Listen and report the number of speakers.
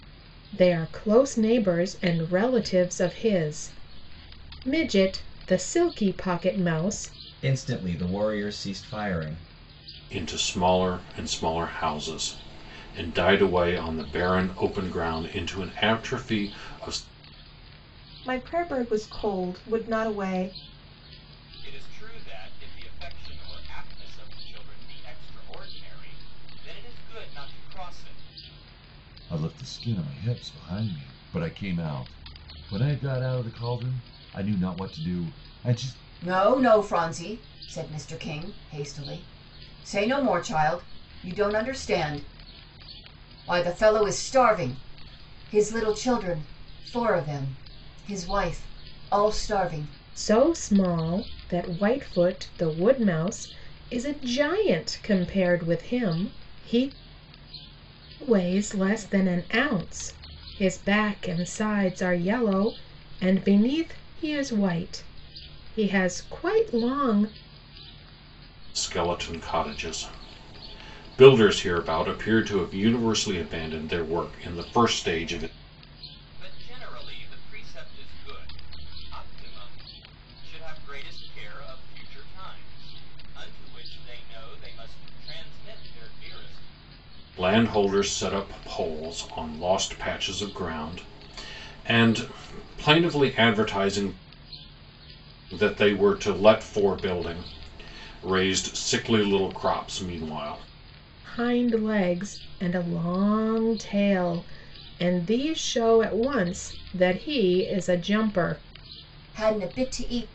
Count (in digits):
7